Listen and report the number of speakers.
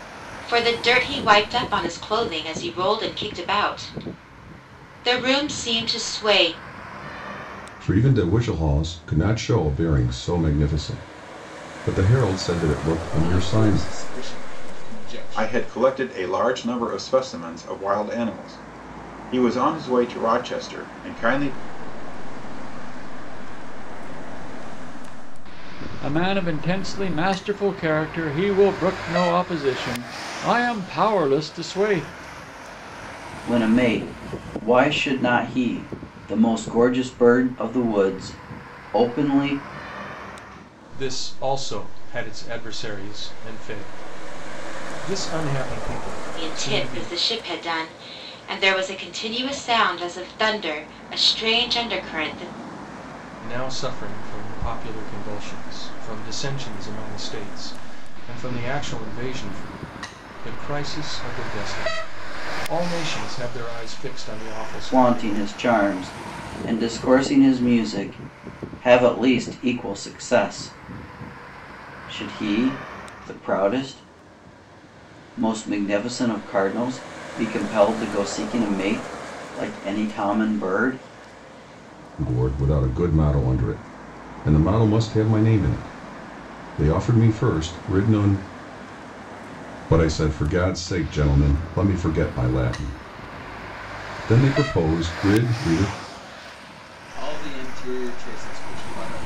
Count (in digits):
8